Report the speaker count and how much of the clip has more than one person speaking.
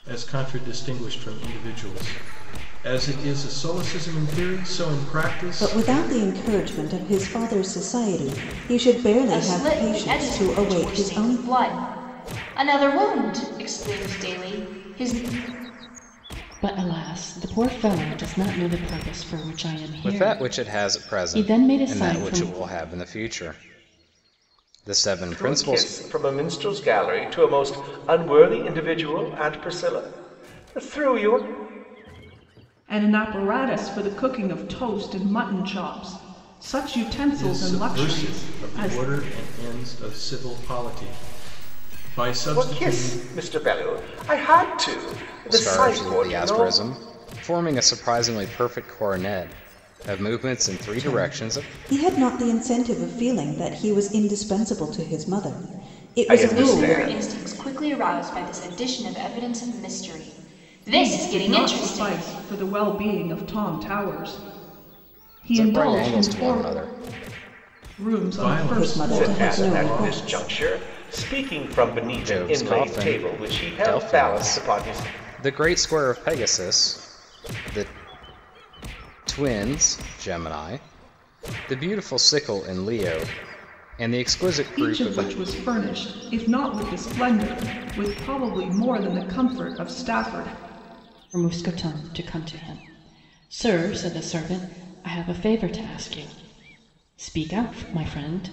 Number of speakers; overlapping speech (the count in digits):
7, about 20%